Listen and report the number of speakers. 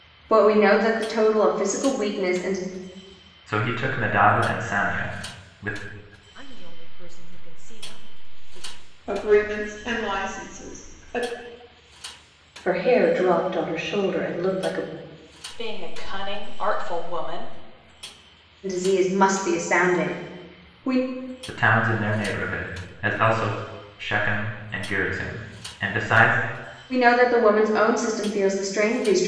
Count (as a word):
six